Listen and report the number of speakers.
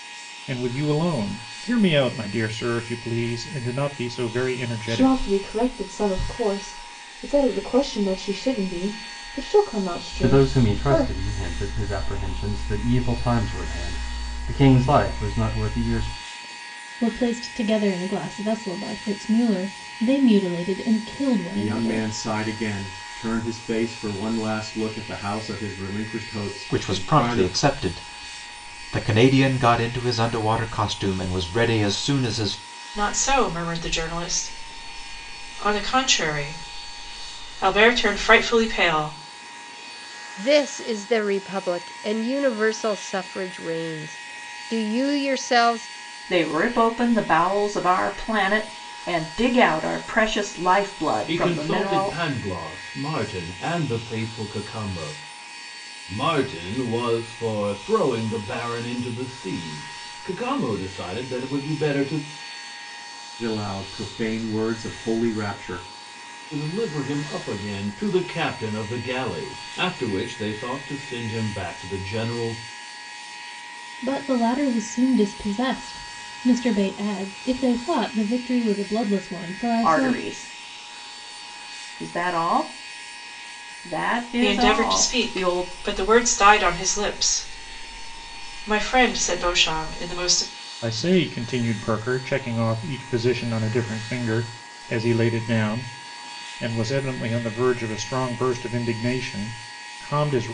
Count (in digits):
10